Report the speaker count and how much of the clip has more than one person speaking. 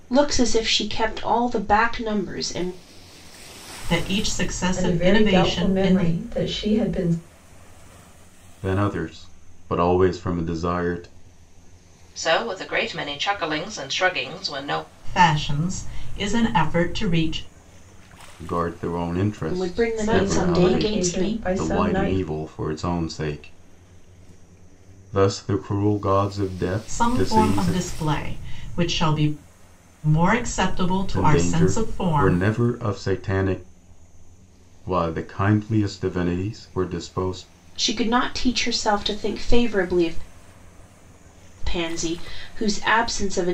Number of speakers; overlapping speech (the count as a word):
five, about 14%